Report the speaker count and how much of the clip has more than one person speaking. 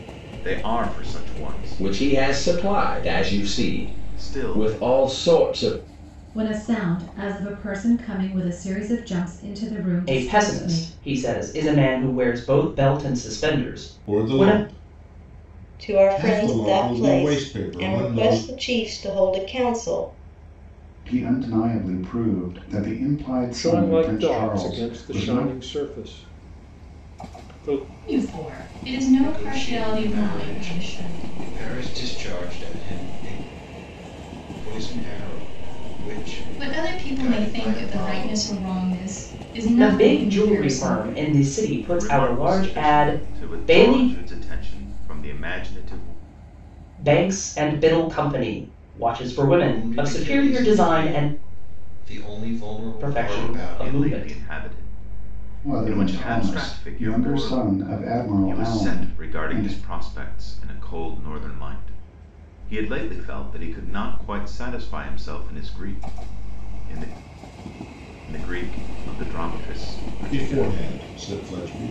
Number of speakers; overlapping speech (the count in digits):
10, about 33%